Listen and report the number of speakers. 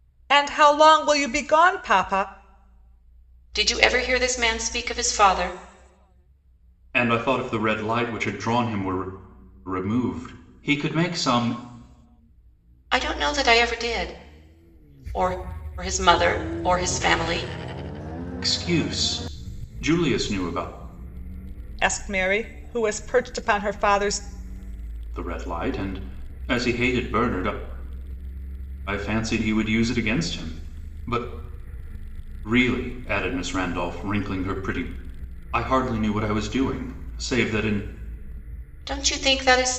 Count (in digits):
3